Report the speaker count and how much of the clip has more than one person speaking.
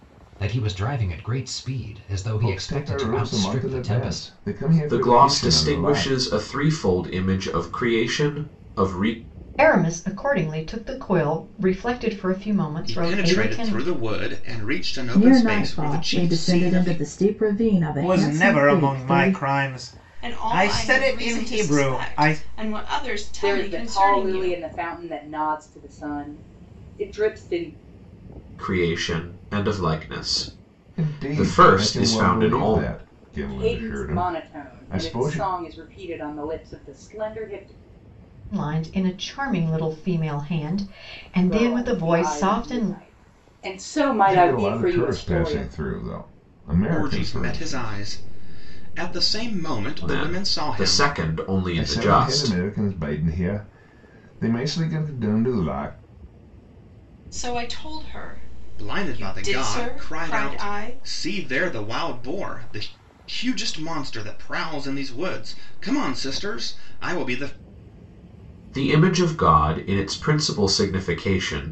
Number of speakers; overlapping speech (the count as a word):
nine, about 33%